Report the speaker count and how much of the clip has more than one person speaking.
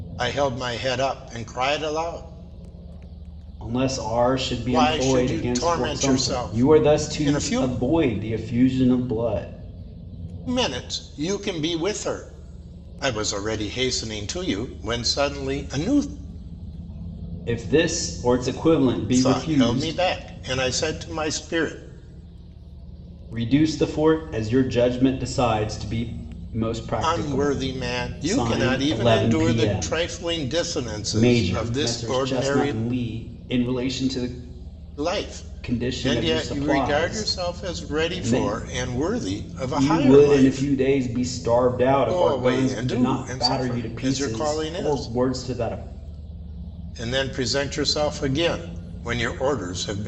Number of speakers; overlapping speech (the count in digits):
2, about 33%